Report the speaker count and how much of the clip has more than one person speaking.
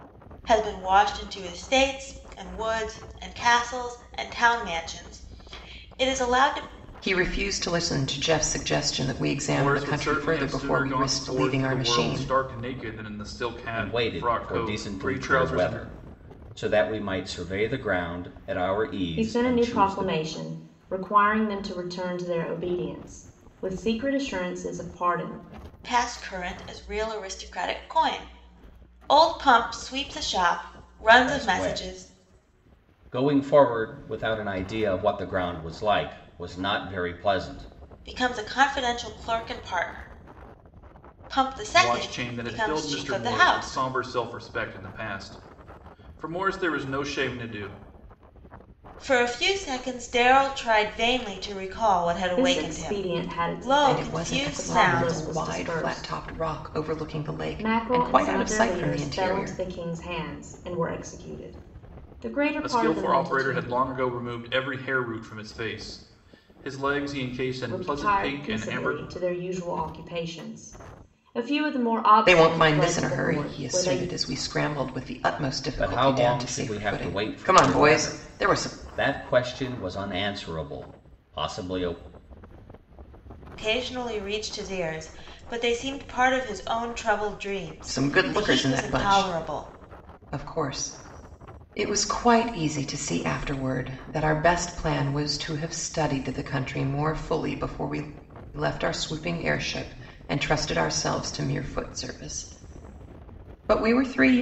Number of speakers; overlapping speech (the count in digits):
5, about 23%